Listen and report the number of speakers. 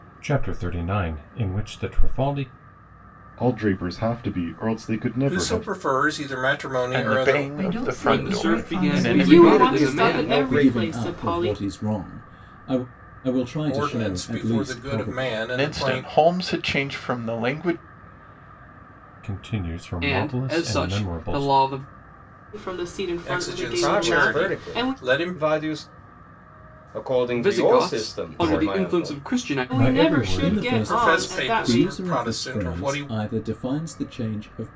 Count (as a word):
nine